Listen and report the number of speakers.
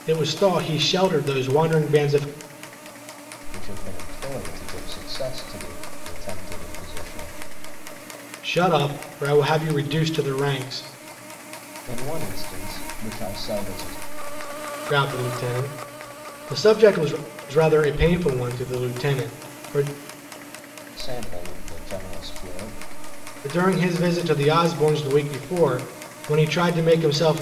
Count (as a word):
two